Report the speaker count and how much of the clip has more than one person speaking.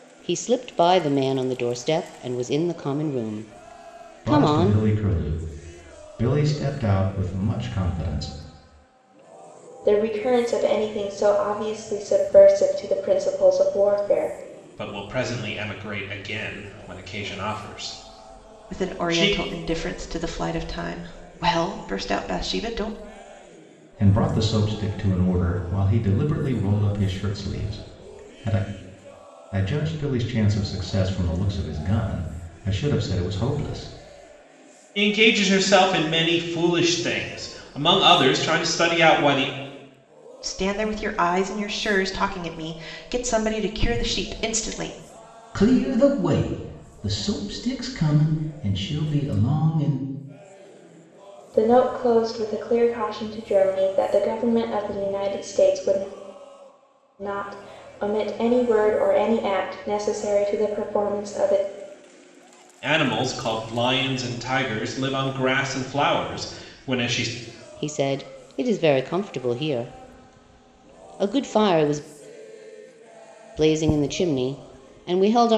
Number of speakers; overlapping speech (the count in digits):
5, about 2%